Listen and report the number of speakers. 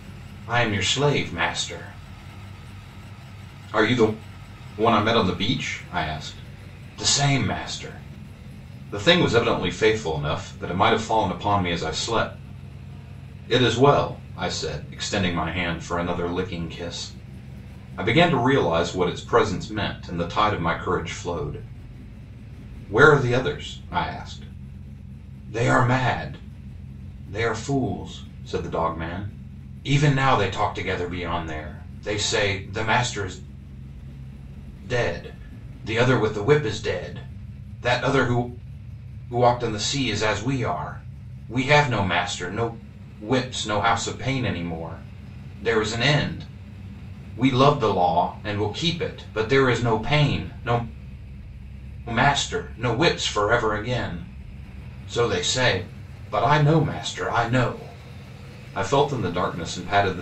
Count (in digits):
1